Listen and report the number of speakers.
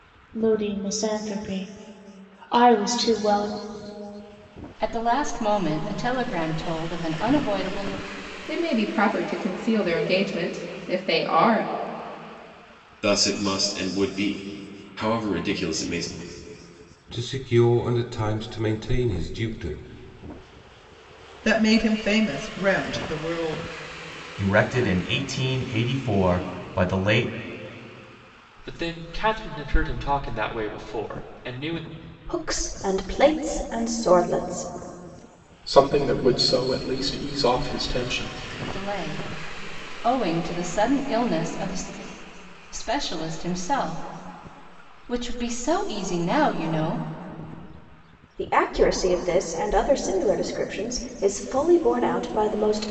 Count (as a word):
ten